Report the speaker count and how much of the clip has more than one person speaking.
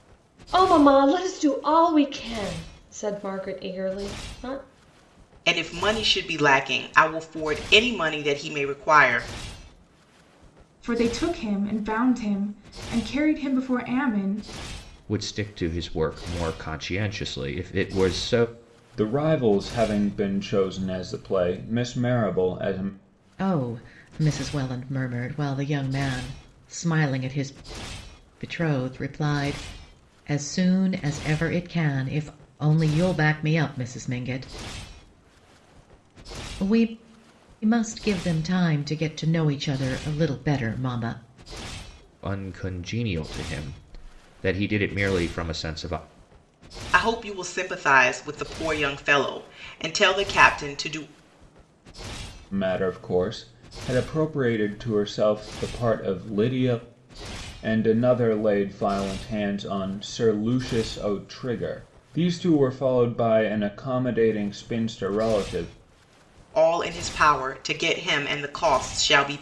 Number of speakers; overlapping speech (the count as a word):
six, no overlap